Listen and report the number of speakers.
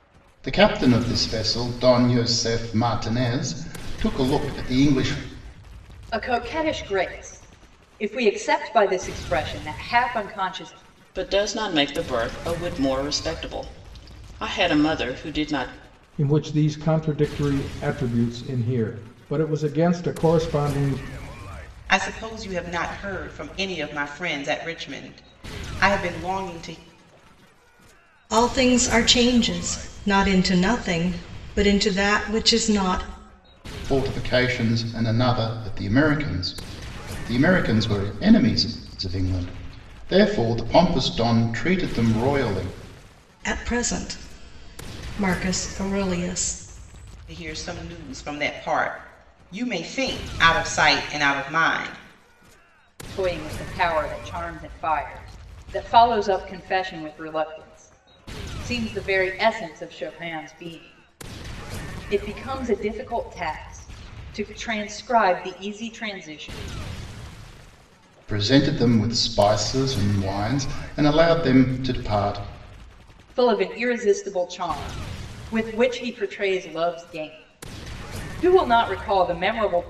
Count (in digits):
6